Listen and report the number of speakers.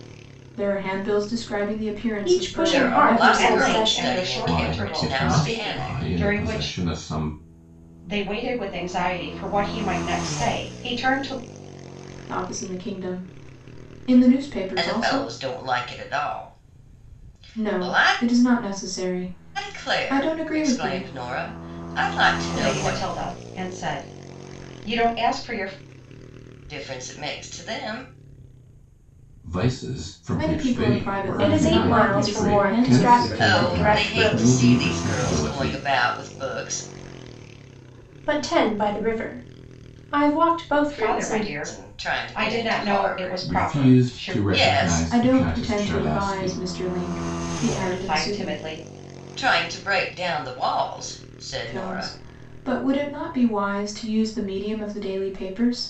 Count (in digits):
5